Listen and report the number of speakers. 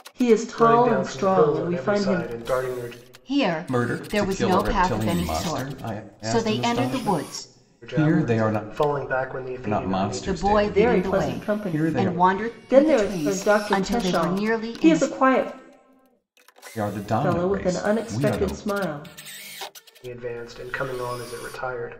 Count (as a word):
four